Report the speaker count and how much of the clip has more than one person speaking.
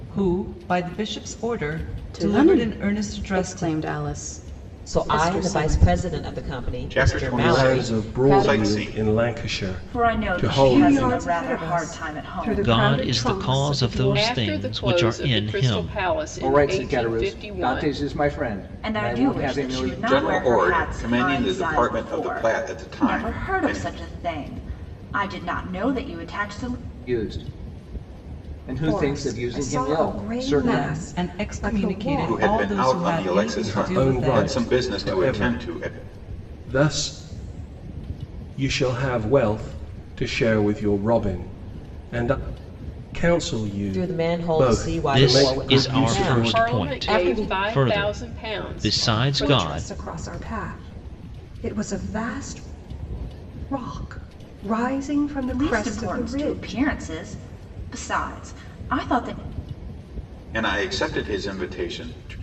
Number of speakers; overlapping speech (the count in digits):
10, about 50%